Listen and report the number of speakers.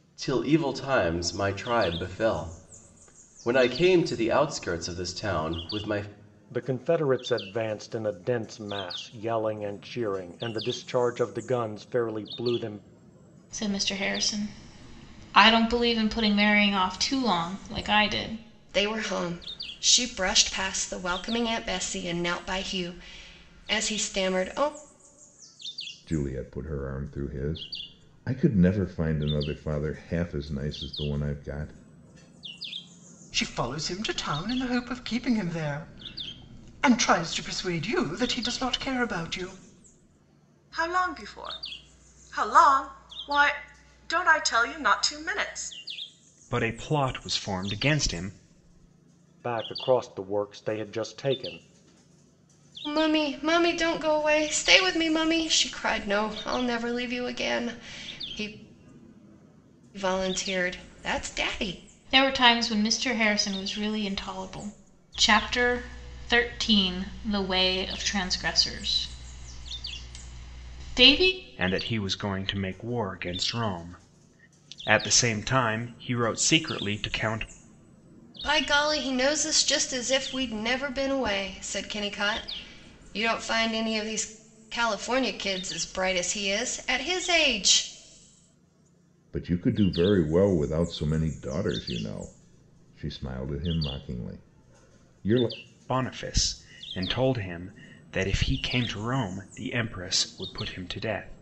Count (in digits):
8